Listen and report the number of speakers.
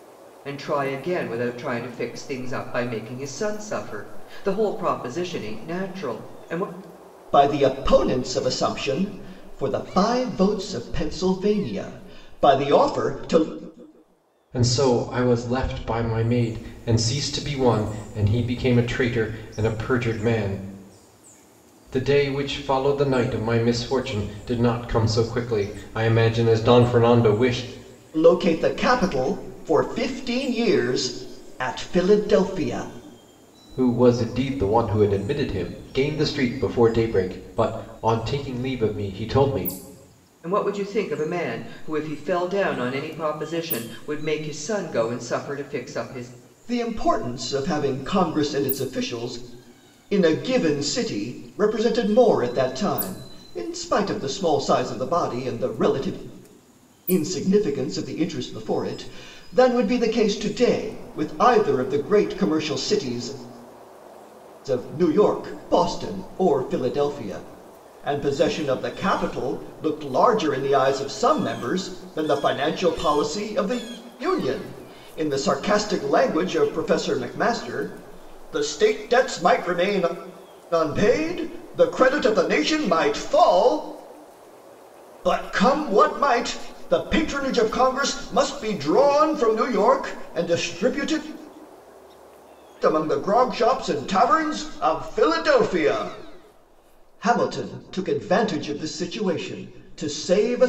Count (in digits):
3